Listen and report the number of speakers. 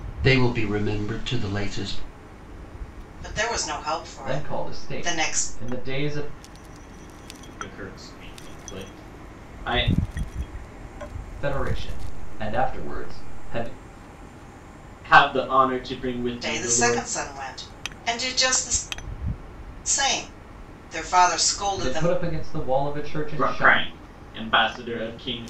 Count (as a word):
four